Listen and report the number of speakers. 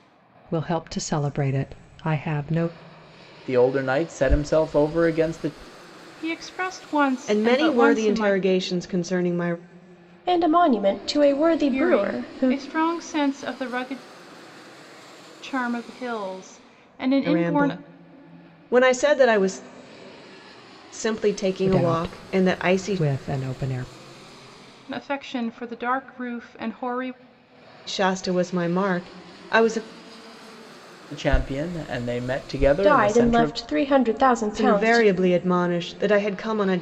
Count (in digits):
5